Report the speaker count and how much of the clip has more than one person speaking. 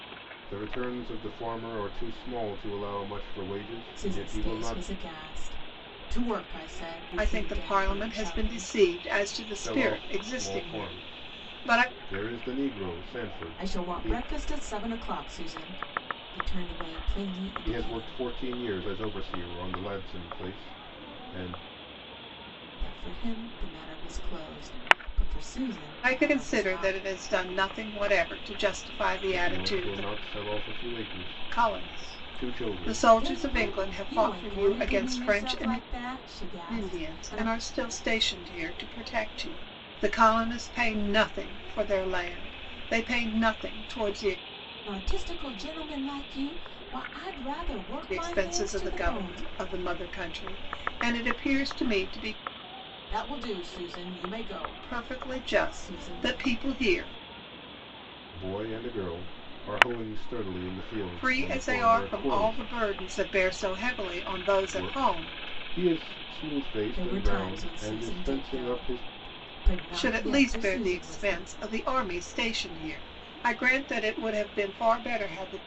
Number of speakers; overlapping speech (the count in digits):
3, about 30%